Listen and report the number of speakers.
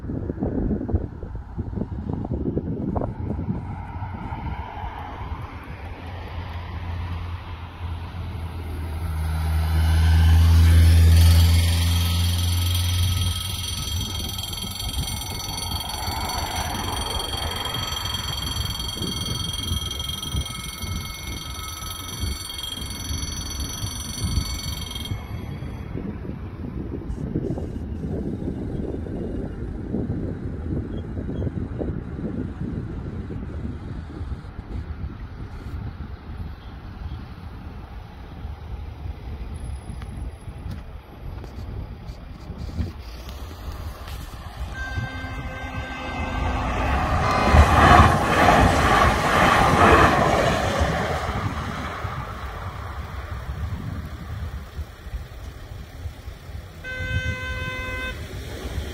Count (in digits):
0